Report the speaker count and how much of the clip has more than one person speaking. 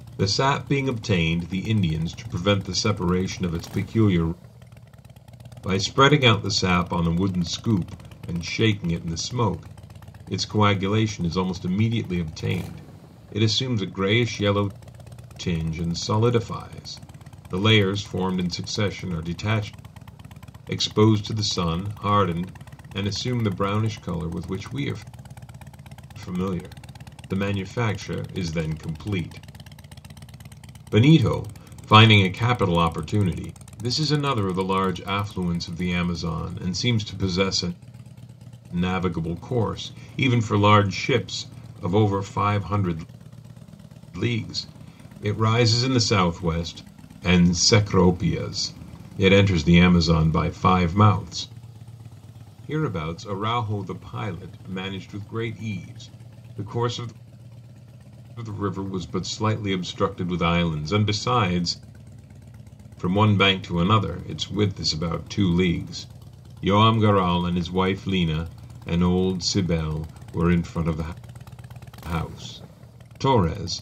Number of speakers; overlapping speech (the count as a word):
one, no overlap